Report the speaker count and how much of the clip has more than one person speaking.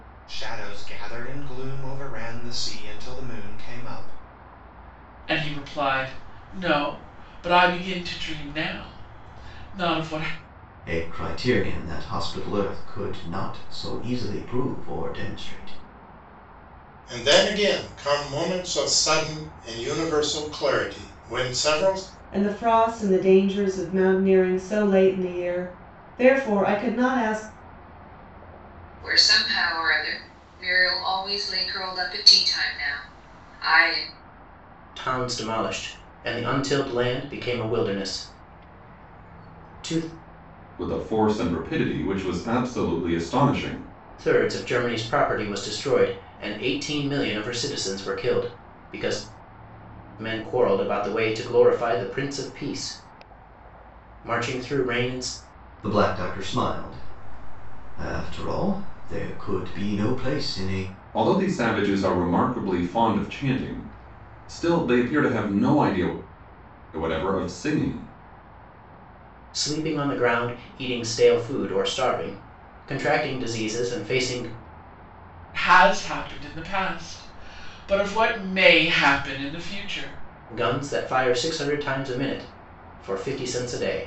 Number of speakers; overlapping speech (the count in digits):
8, no overlap